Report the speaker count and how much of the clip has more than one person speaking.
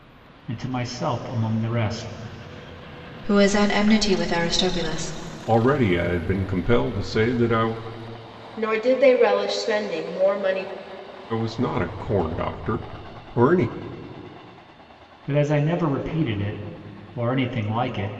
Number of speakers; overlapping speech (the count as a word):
four, no overlap